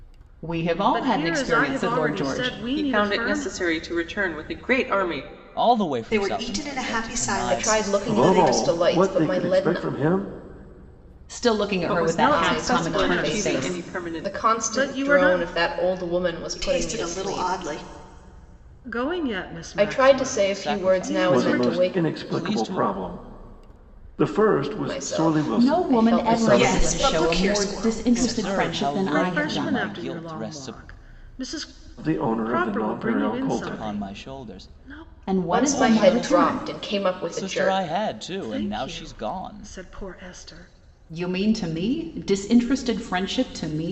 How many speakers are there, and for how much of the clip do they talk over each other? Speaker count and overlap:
seven, about 59%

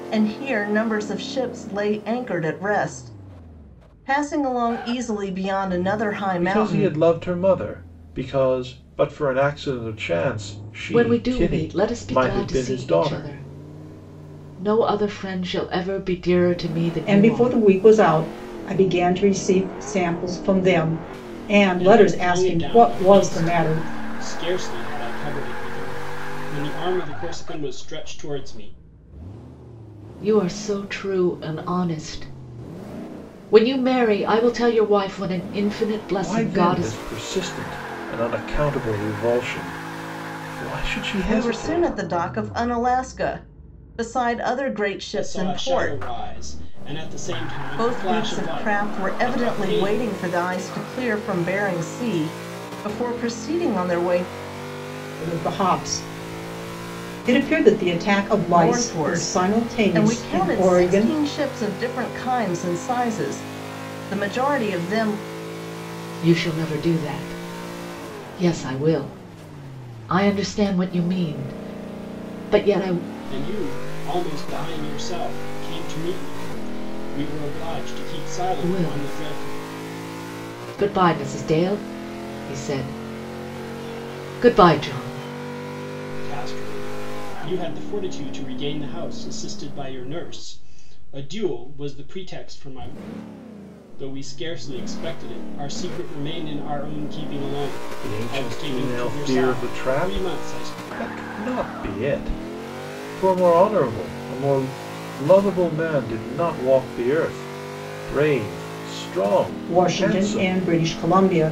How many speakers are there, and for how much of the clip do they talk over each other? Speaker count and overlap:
five, about 16%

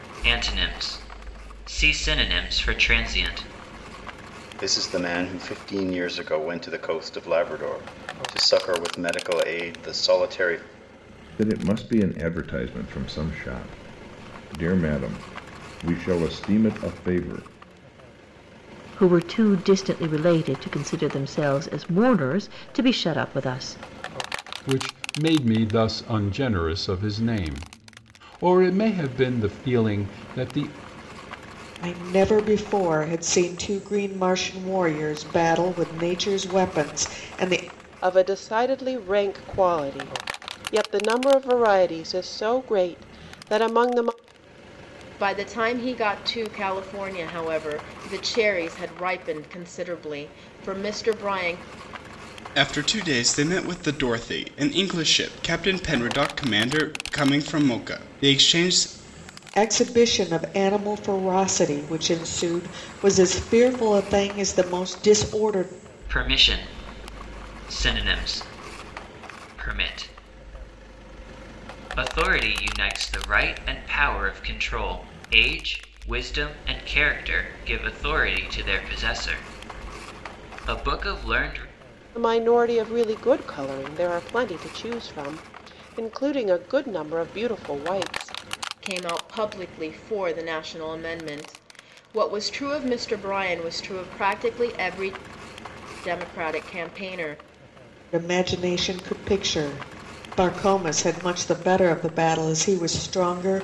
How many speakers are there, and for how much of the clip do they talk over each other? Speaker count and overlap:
nine, no overlap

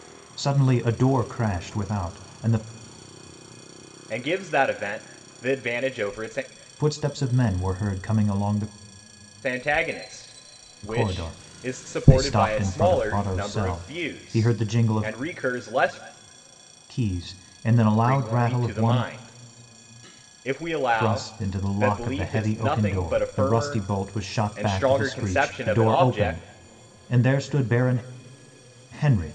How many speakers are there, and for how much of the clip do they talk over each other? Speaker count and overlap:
two, about 35%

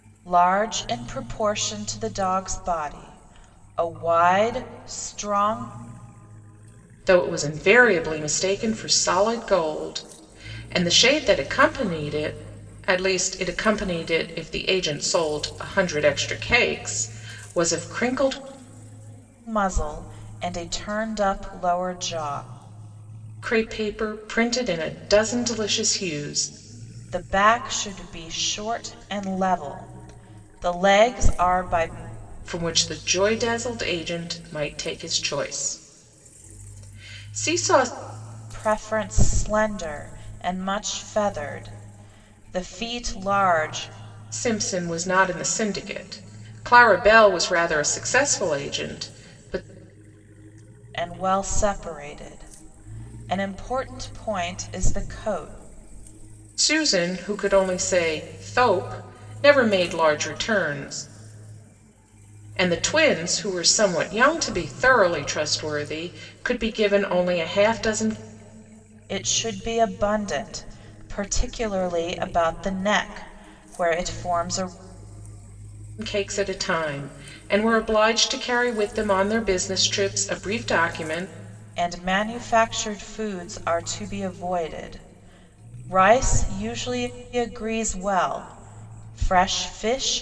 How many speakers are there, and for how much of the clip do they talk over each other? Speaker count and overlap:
two, no overlap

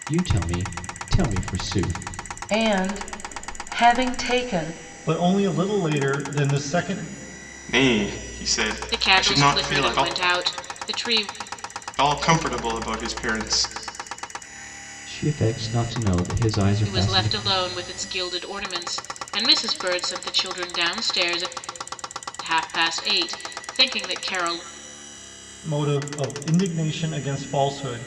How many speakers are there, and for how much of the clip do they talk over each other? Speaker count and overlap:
five, about 6%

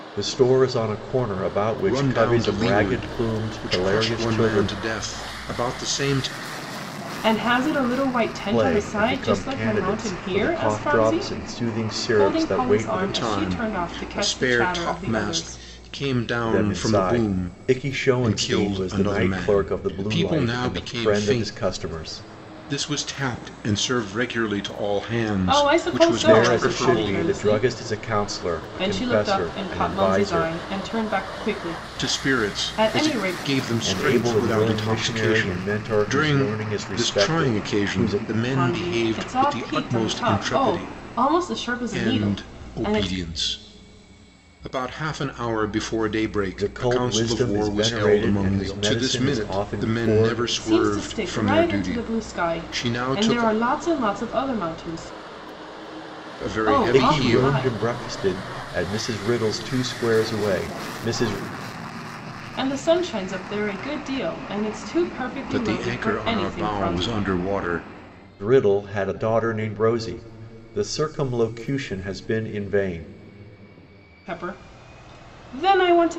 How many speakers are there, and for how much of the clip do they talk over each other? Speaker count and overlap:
three, about 48%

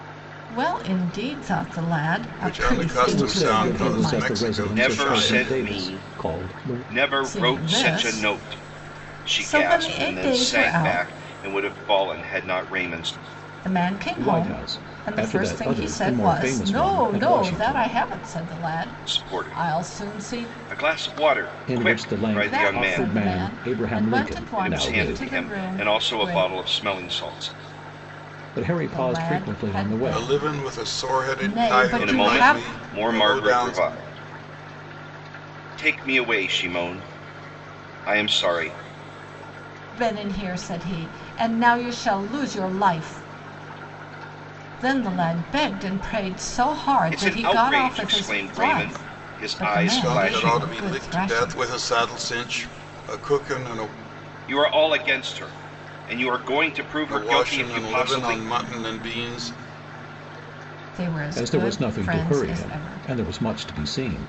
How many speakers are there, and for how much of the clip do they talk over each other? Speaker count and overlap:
four, about 47%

